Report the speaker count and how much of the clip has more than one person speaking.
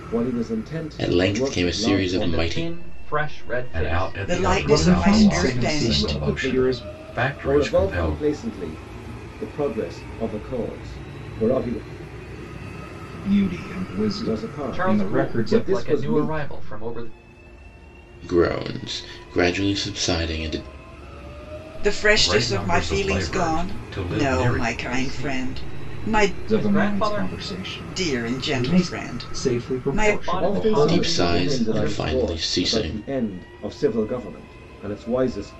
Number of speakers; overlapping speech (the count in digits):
6, about 50%